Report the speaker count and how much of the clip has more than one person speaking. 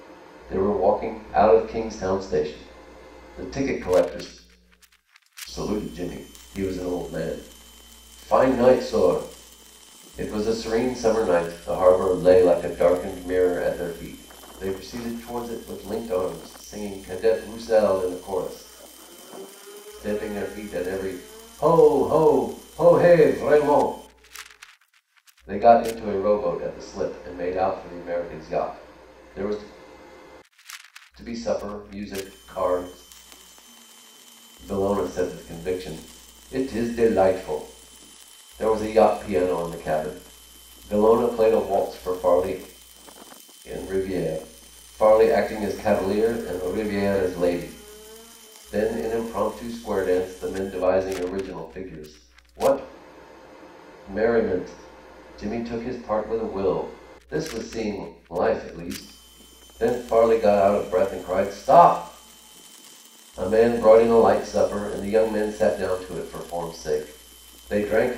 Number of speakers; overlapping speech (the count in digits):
1, no overlap